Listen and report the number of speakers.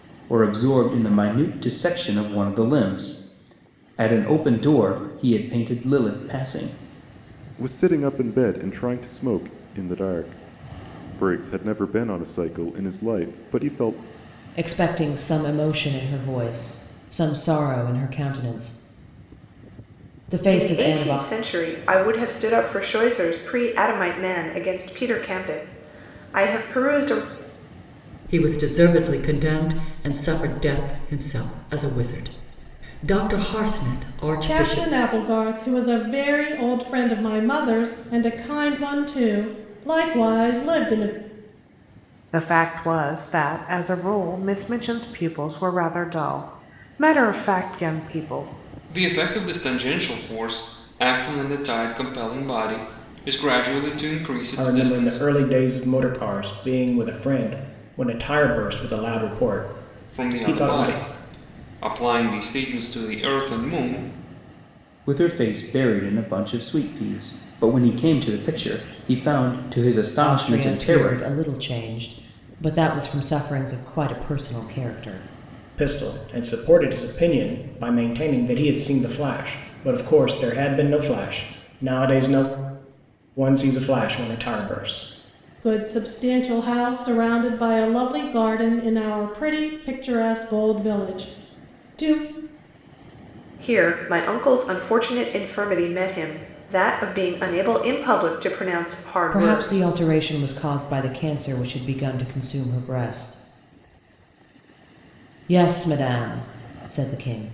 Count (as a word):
nine